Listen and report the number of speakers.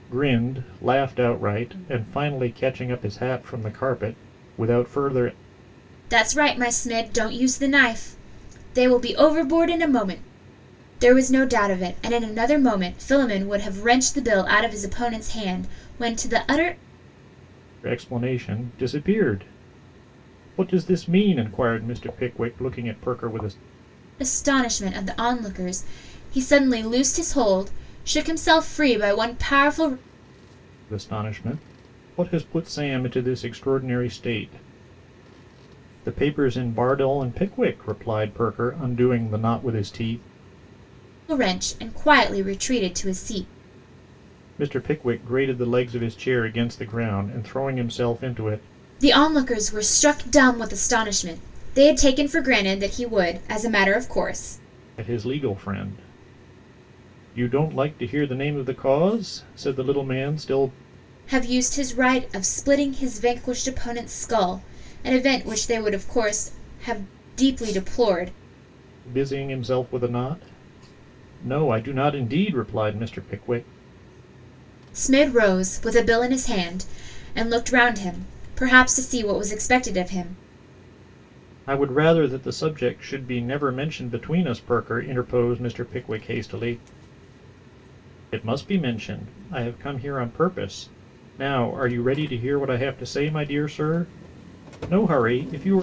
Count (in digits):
2